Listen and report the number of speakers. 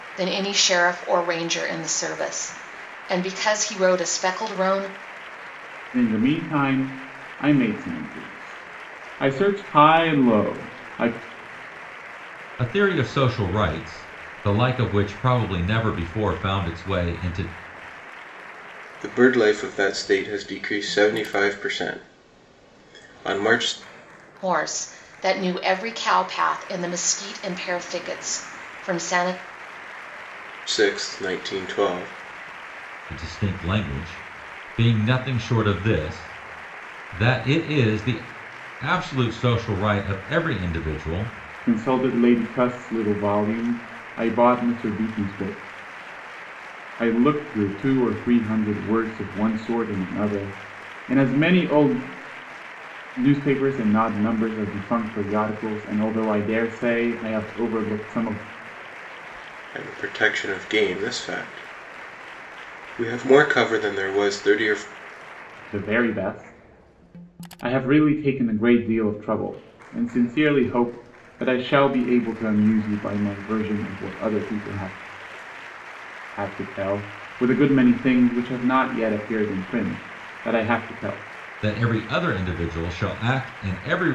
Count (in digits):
4